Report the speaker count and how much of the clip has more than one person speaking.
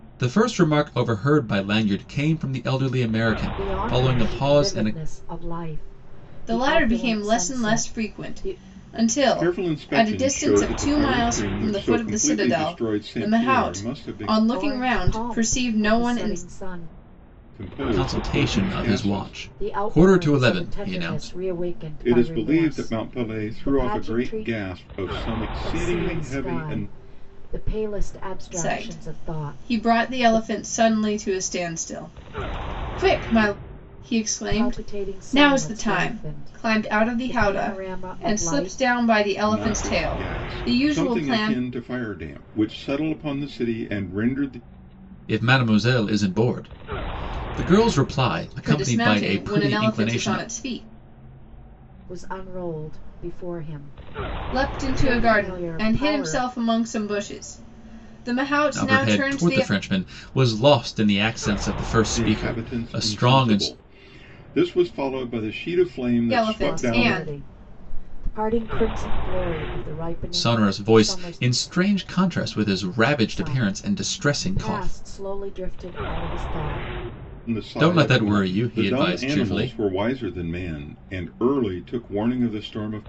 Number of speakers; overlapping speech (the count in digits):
4, about 46%